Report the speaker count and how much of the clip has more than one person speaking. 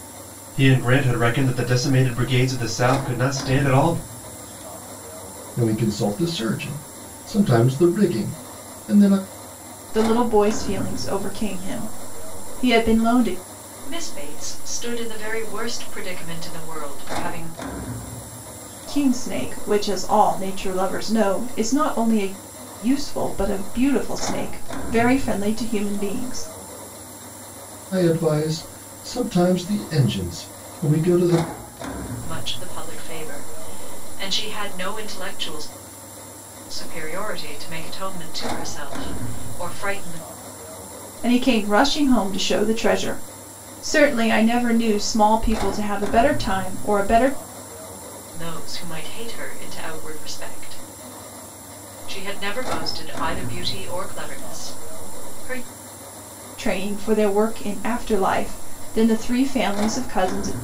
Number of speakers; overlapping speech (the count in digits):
4, no overlap